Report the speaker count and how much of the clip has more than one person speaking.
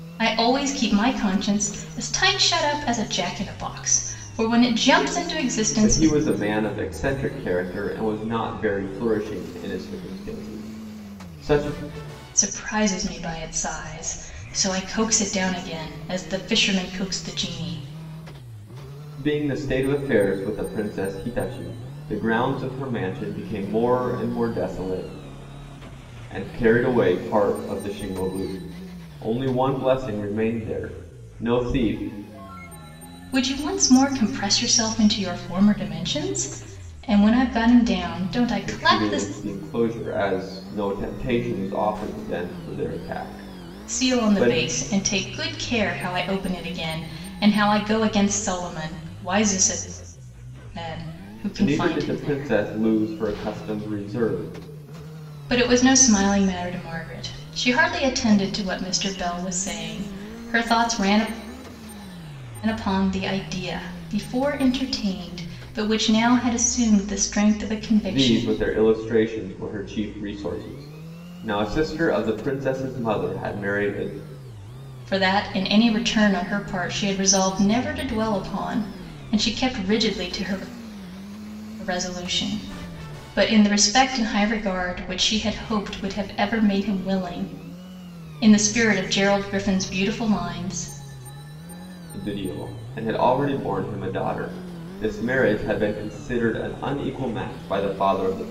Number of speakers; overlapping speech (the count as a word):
two, about 3%